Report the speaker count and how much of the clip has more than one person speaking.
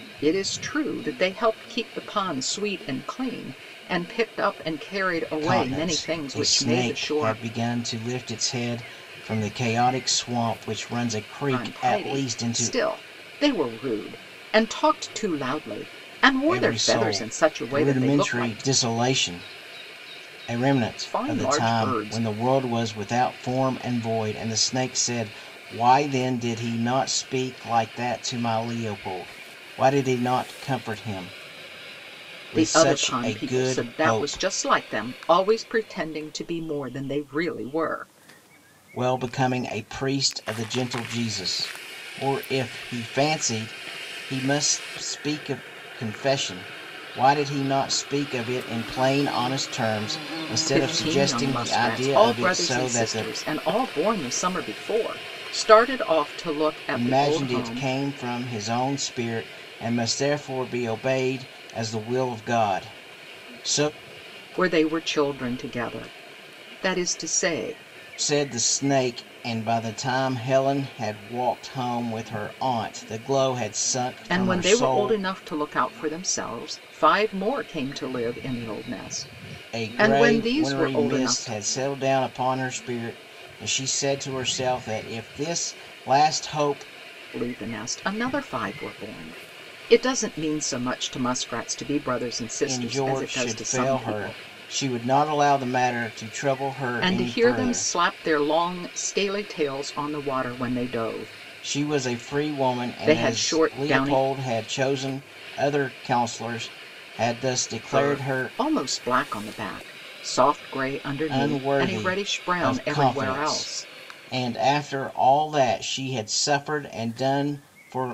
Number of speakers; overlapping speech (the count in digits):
2, about 20%